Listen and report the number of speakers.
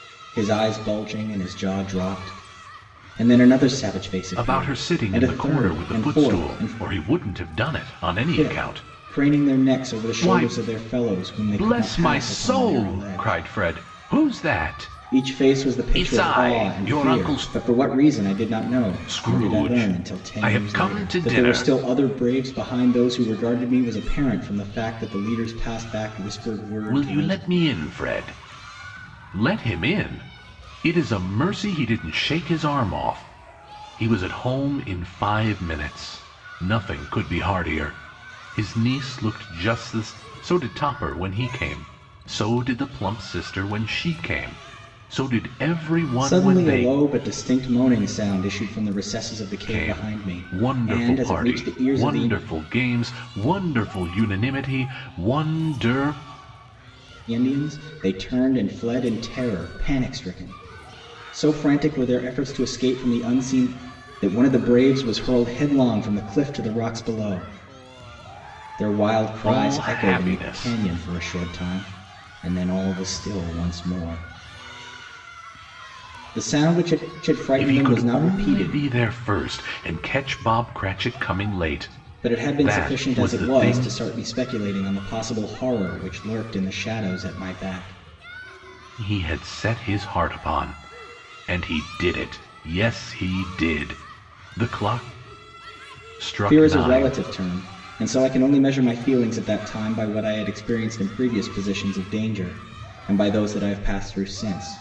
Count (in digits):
2